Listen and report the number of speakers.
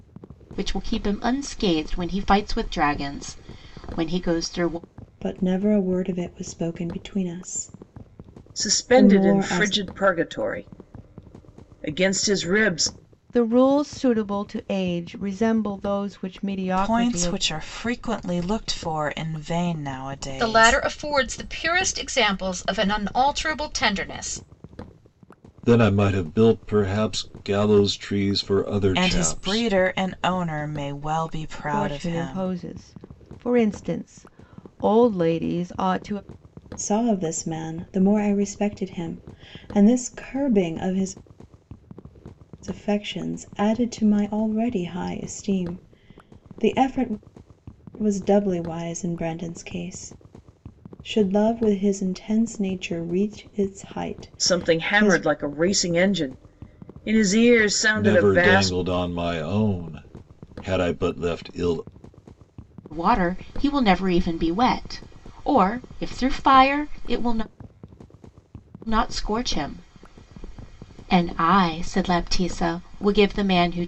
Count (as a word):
seven